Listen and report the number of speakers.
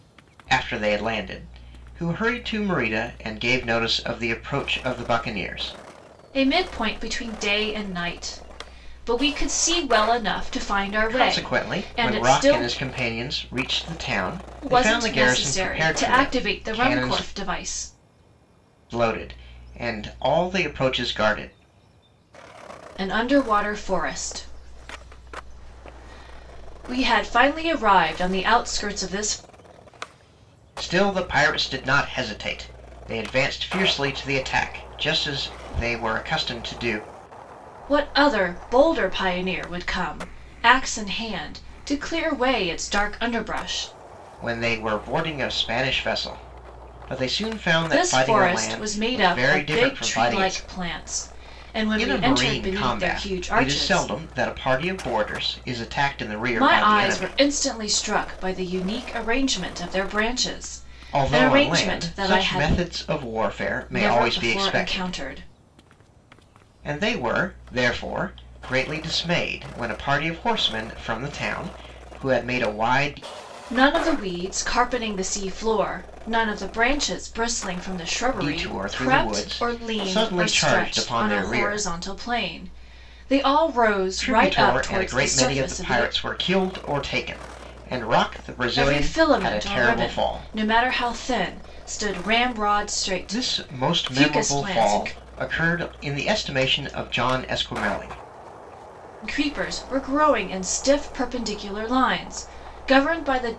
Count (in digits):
2